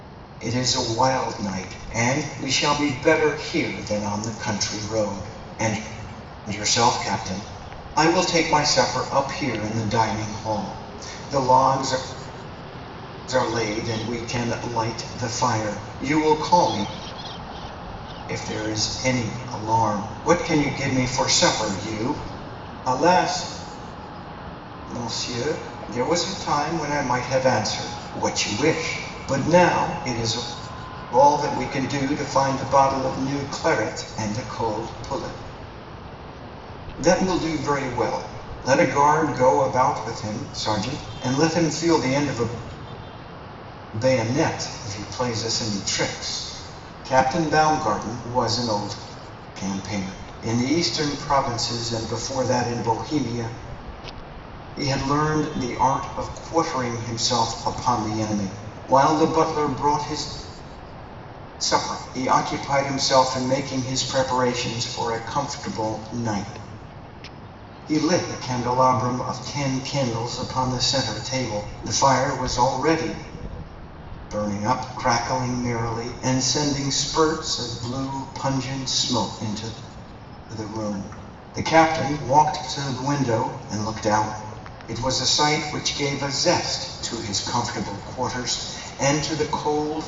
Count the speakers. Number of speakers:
one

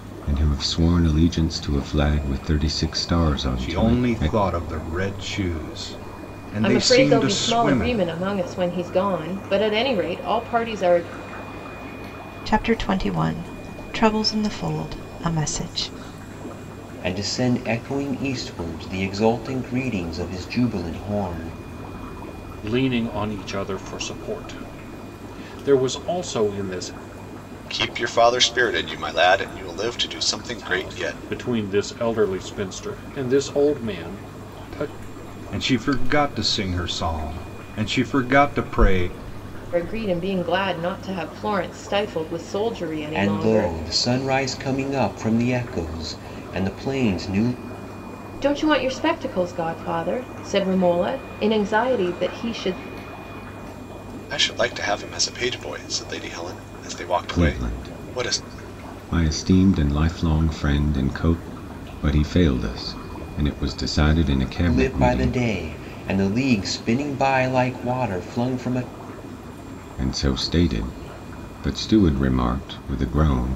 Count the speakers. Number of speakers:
seven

